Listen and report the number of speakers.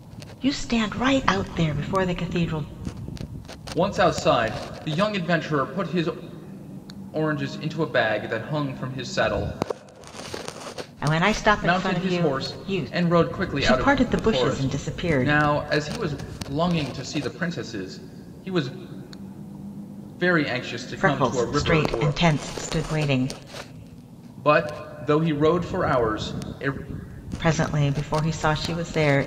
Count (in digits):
2